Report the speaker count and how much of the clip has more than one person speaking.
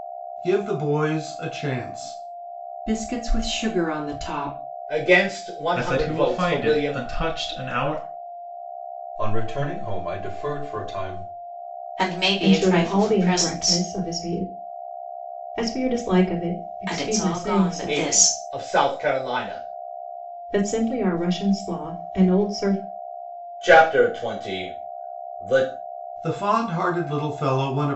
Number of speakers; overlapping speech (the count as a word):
seven, about 15%